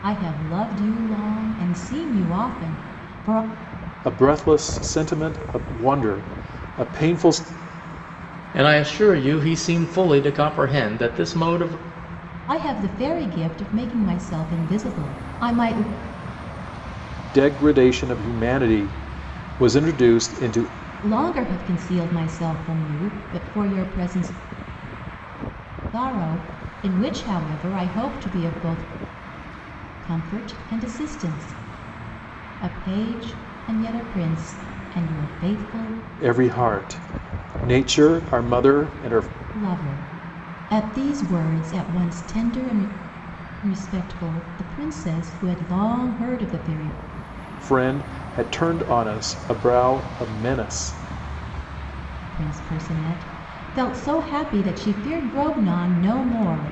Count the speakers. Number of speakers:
3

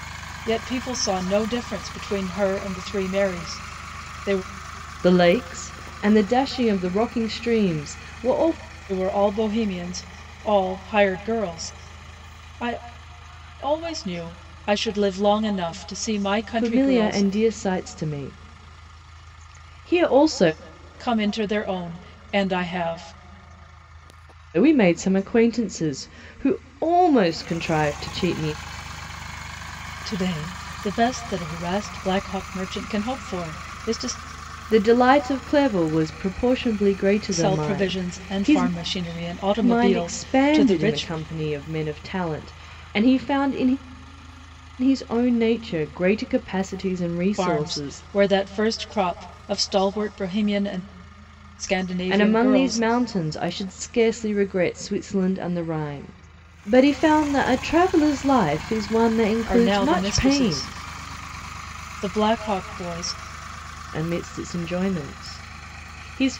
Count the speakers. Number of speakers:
2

